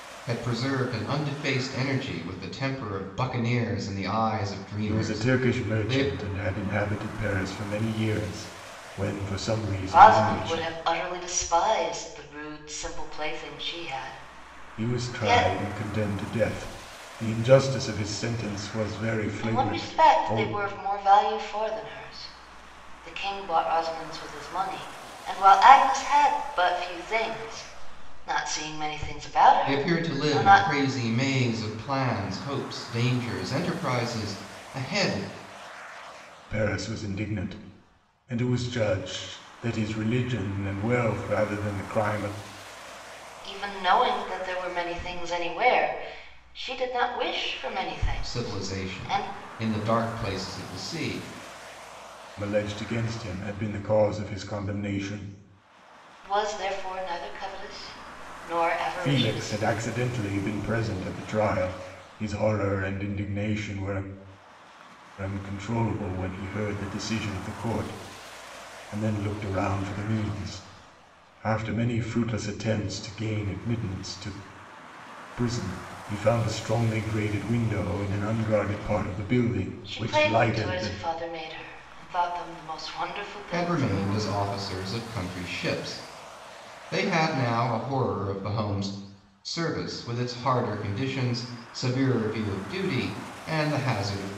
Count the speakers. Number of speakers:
three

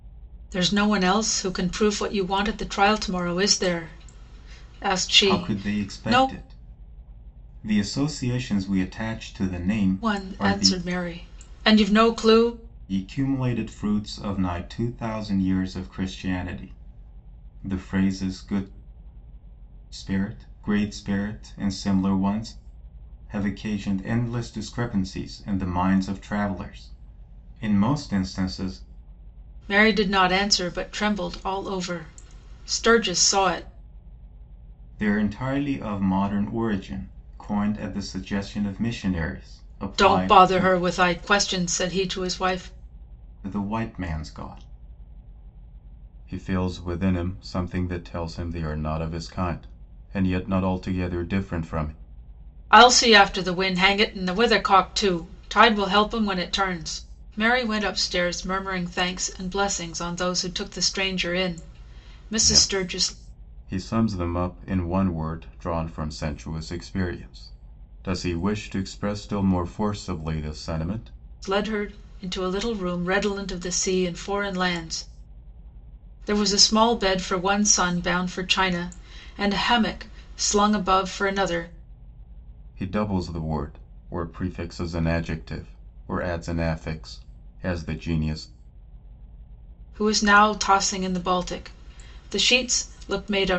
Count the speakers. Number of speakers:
two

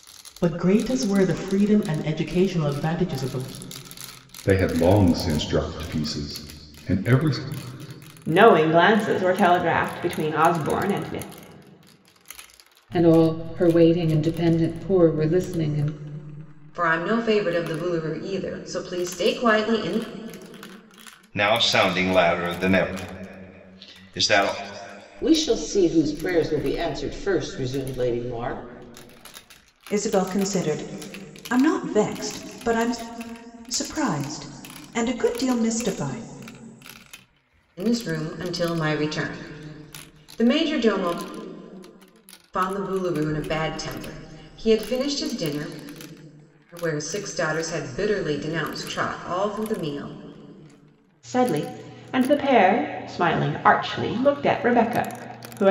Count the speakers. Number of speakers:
eight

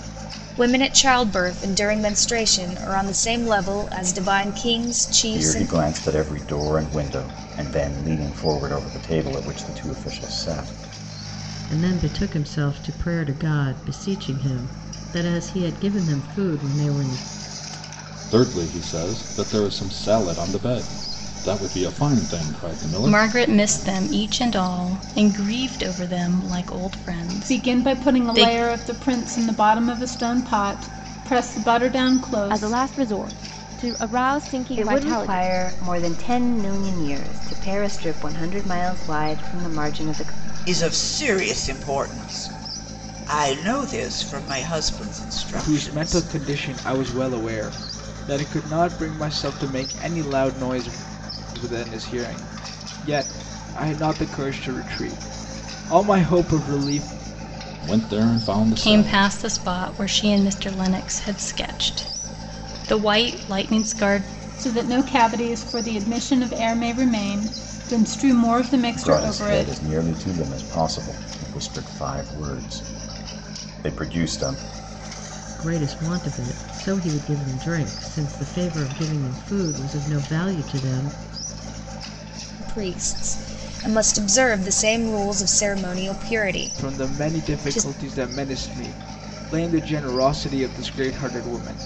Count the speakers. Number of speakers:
ten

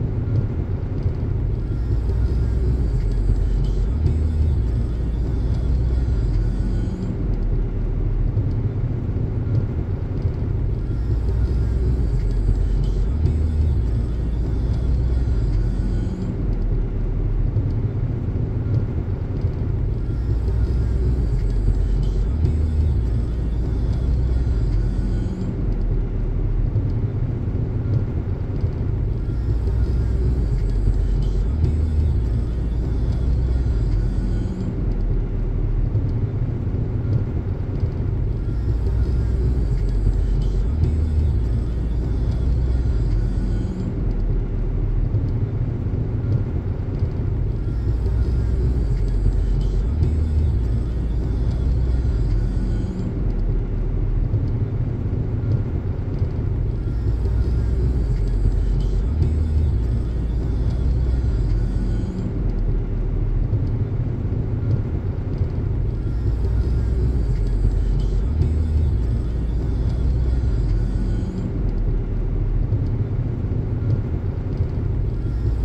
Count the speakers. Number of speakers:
zero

